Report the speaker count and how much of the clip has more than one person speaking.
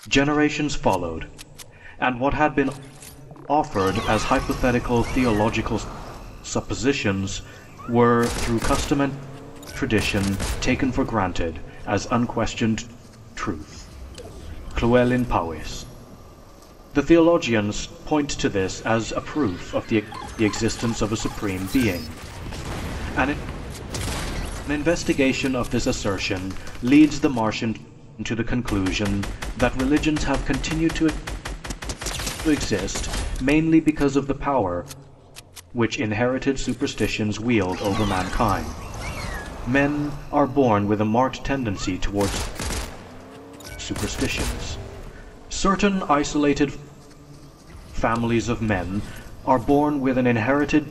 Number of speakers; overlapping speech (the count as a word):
one, no overlap